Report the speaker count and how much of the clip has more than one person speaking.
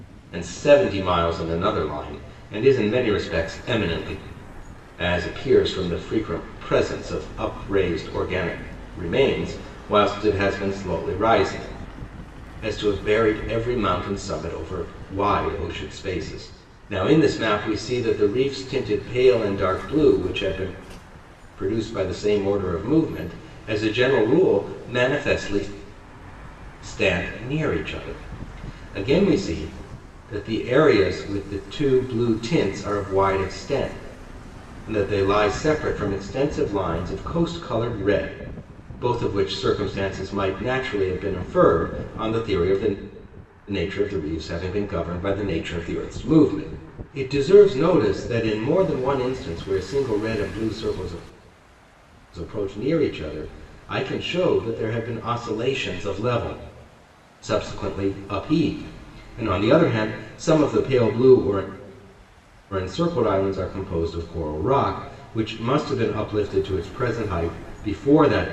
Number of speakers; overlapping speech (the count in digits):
1, no overlap